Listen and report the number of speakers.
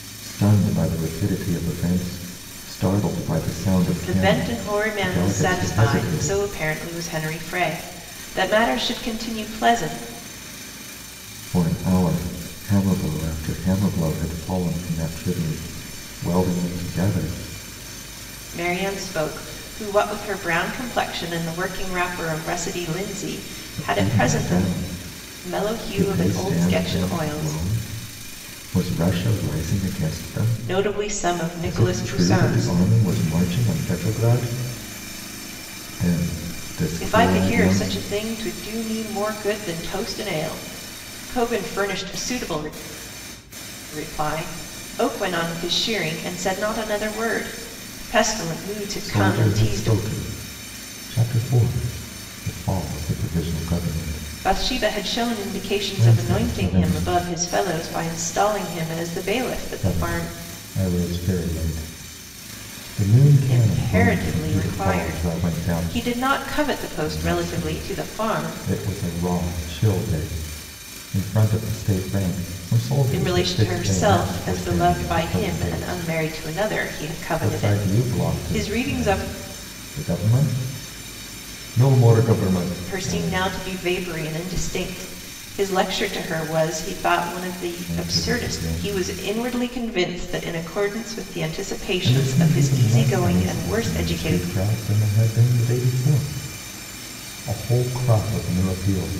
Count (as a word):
two